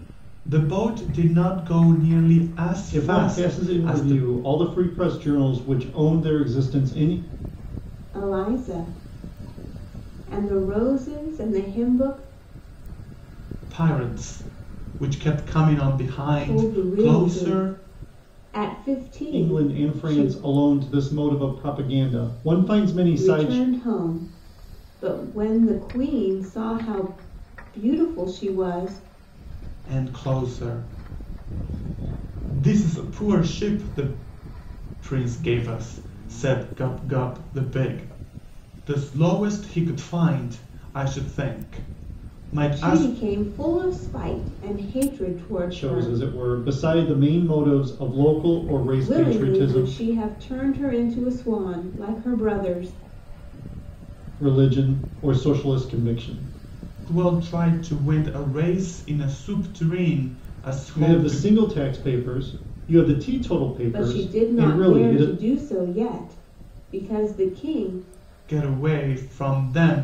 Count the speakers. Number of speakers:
three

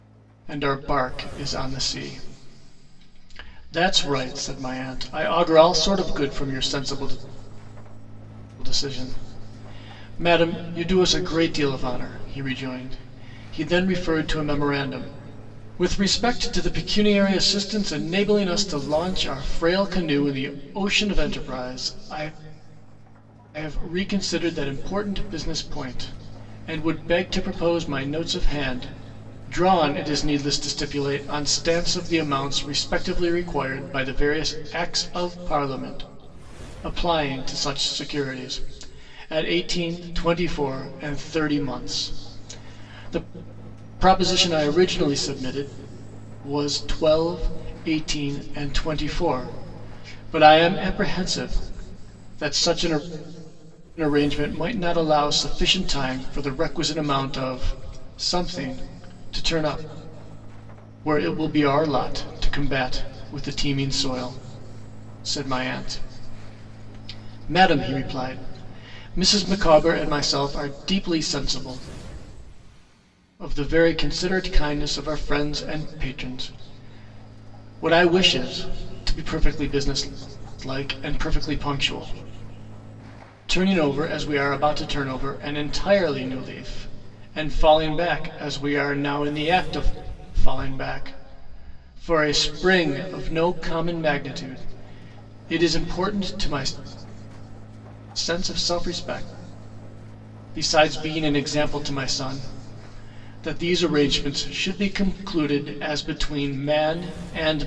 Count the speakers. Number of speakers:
one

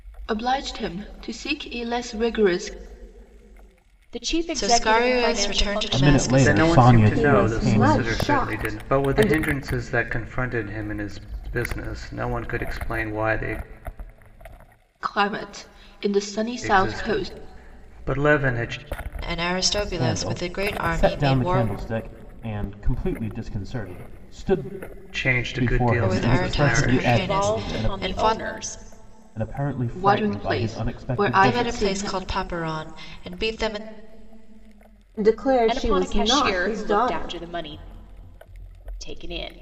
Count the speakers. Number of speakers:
six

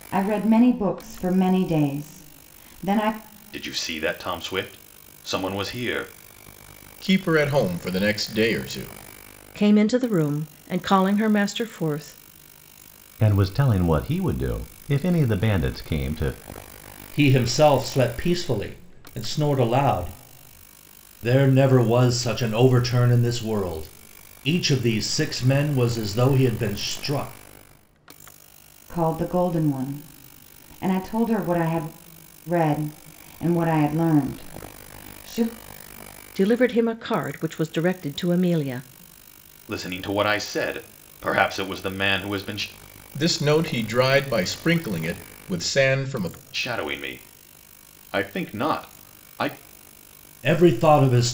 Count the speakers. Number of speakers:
six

